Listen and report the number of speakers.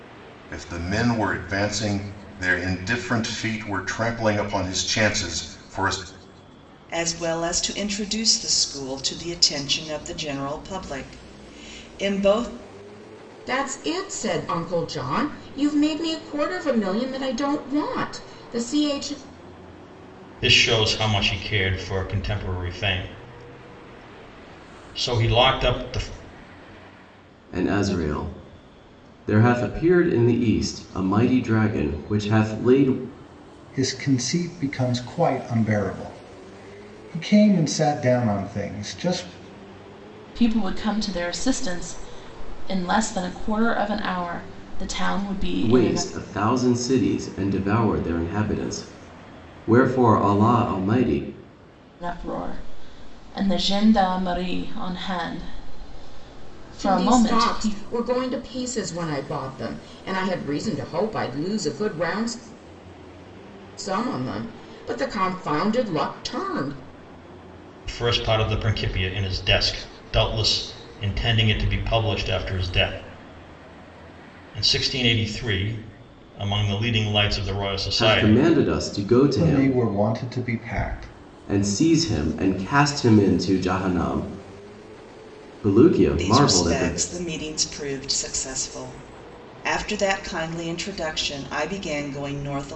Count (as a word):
seven